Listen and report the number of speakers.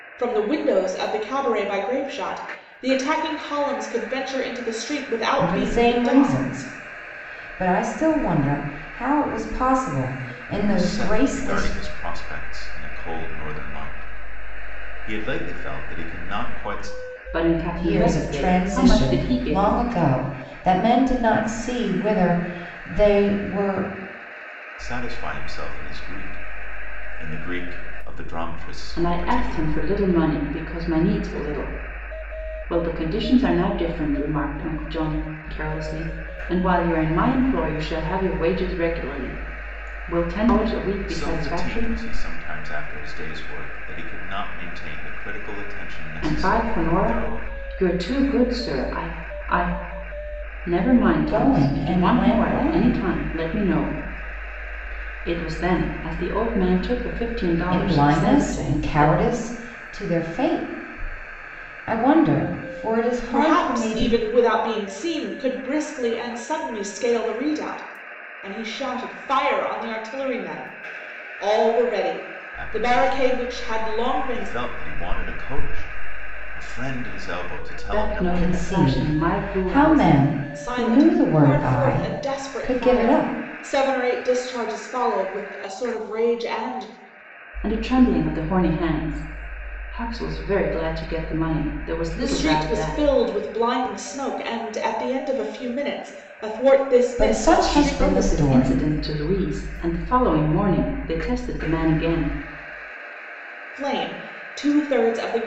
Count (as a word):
four